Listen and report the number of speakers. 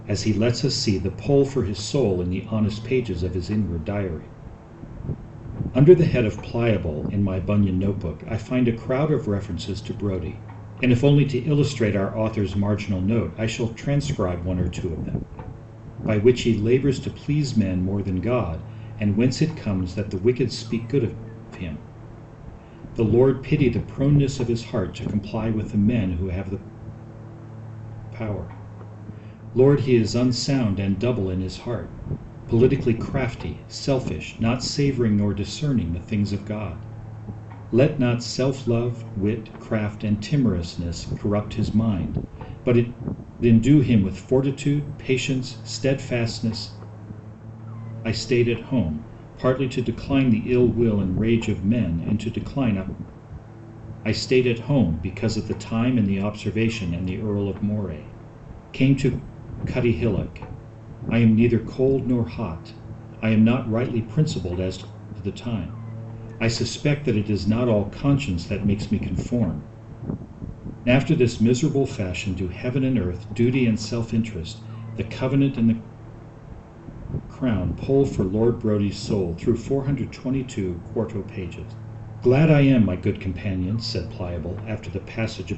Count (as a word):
one